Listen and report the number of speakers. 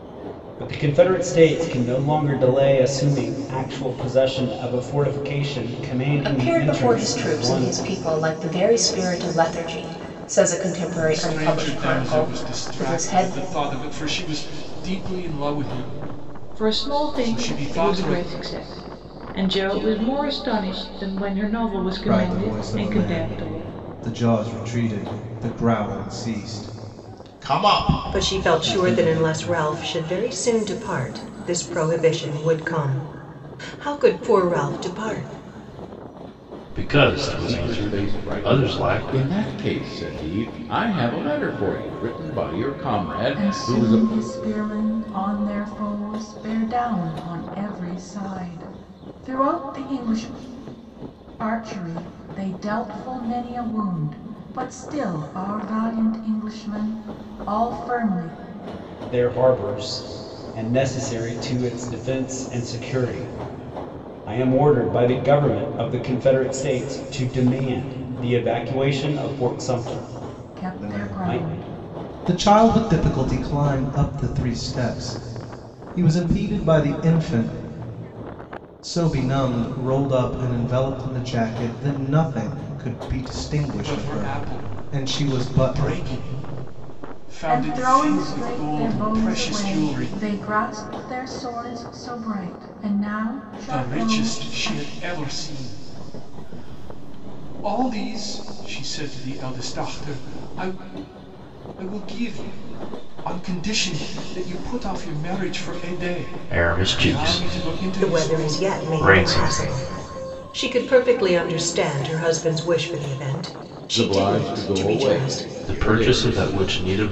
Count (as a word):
nine